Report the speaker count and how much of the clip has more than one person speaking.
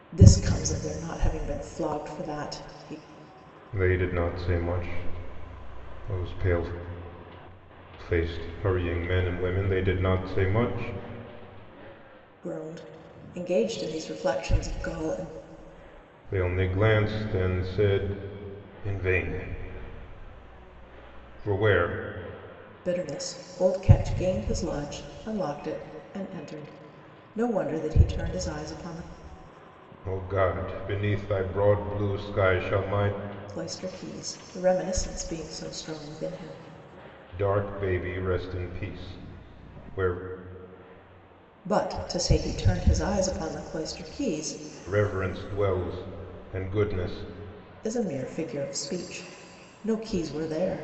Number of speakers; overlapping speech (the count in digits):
2, no overlap